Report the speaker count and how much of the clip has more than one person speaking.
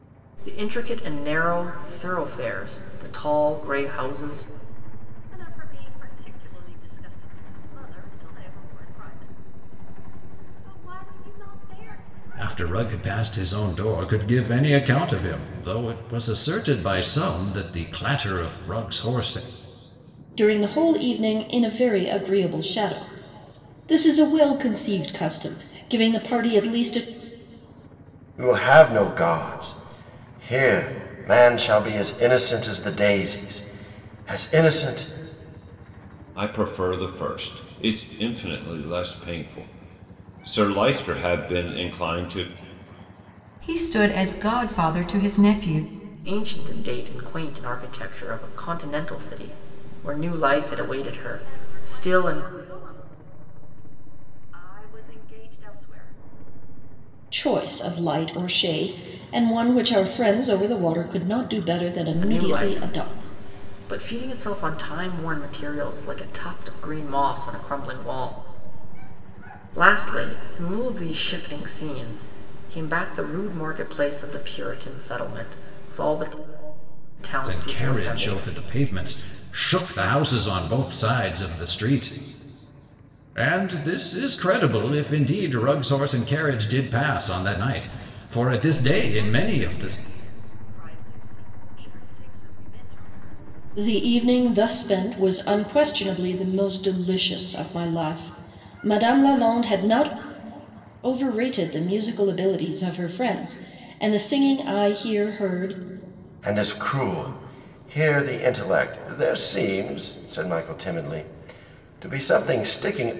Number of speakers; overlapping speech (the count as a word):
seven, about 4%